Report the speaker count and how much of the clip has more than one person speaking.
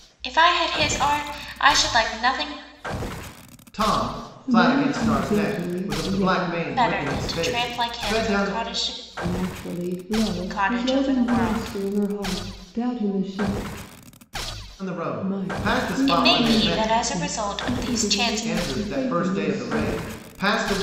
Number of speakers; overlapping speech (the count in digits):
3, about 49%